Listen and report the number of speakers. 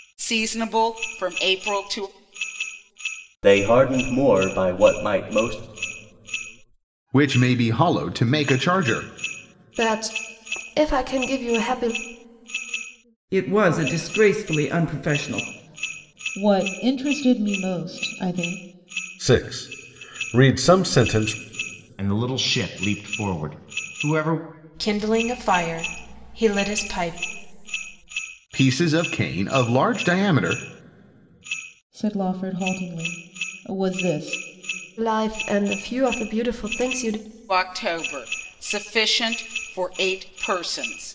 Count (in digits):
9